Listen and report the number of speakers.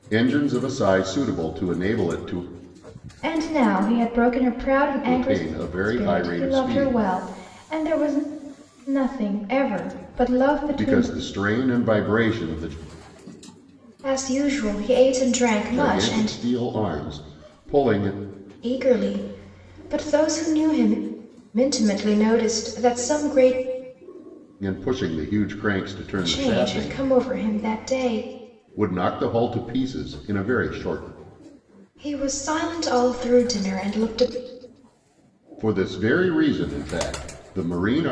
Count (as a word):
two